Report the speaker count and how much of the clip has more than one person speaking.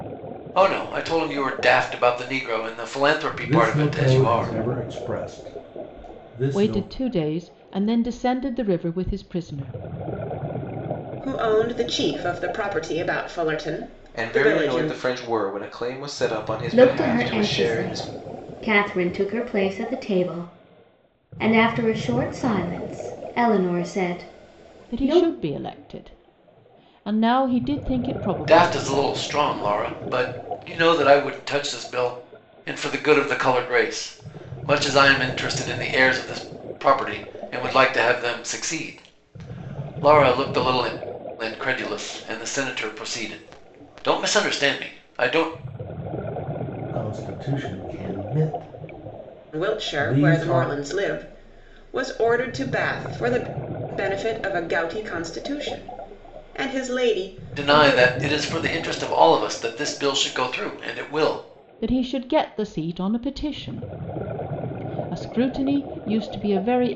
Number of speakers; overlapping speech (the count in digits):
6, about 10%